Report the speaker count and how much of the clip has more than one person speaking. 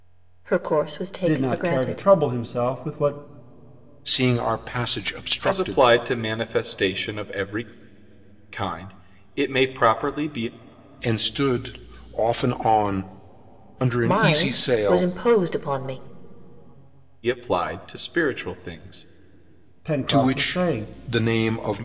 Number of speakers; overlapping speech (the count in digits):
4, about 15%